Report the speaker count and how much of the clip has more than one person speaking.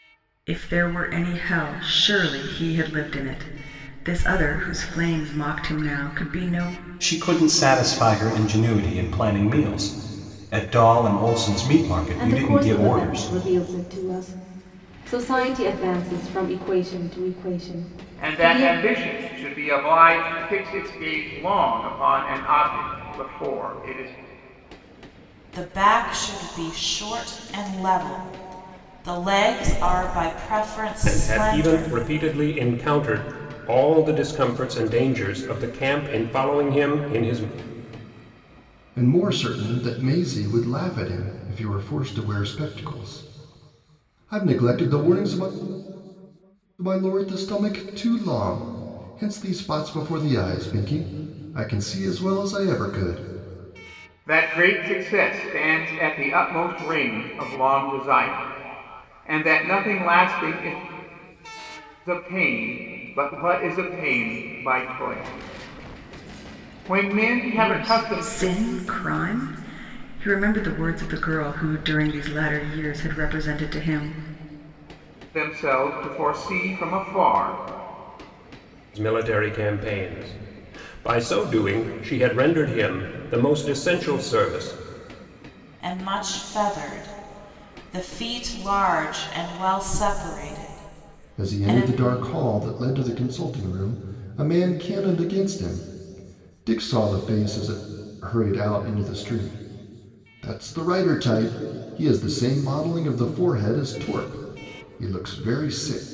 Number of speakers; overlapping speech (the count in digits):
7, about 4%